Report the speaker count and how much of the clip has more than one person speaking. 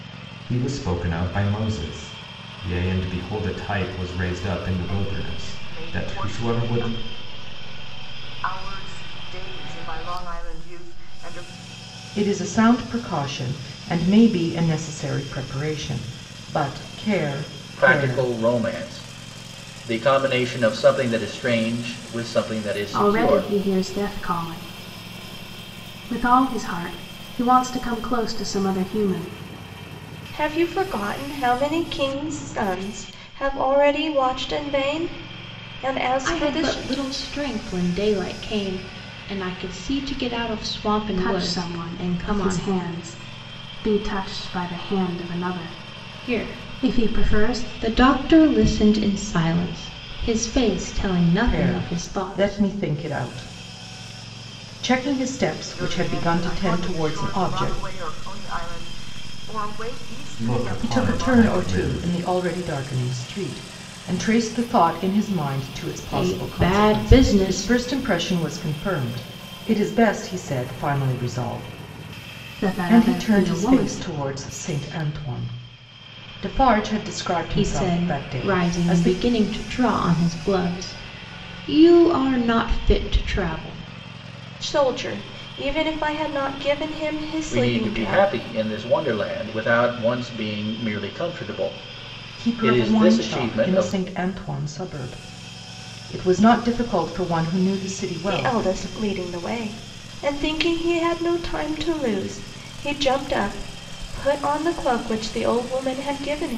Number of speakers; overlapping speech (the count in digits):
7, about 19%